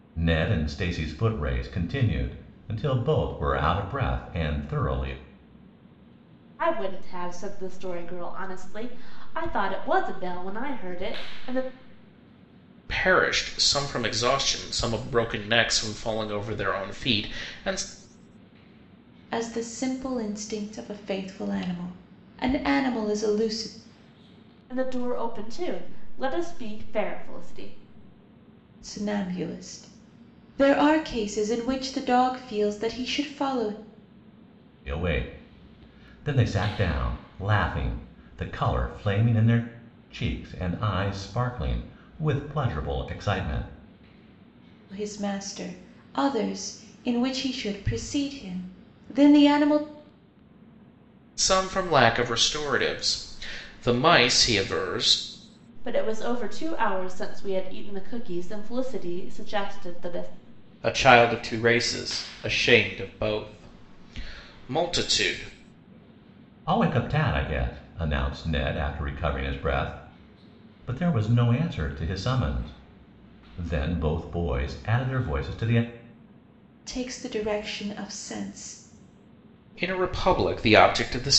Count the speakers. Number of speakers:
four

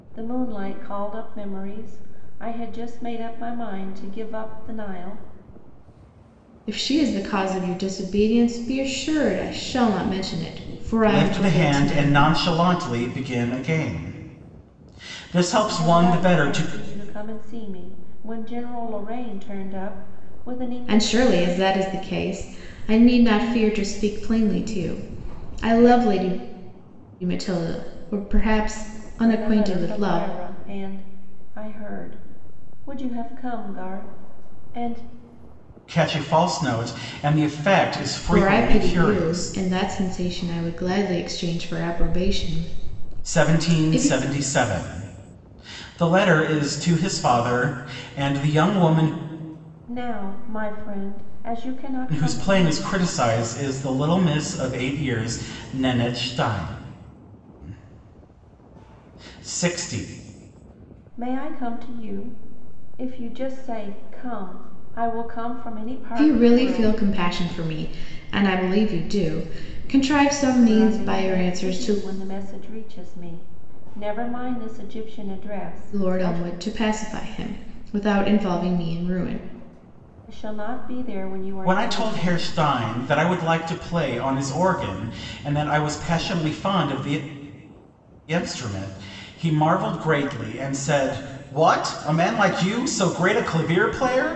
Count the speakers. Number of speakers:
three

